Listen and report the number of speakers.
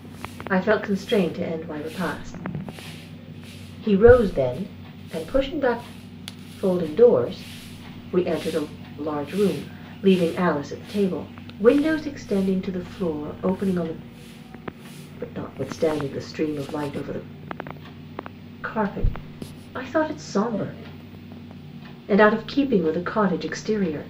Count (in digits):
1